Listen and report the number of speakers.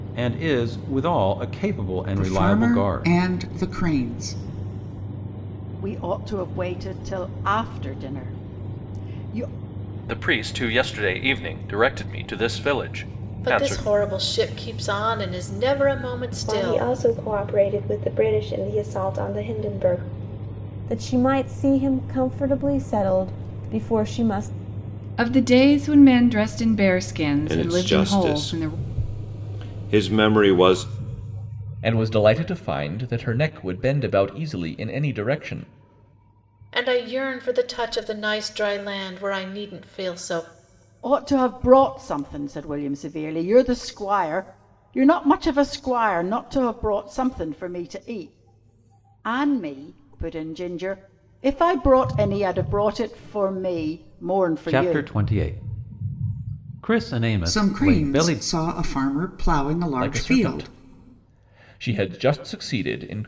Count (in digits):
10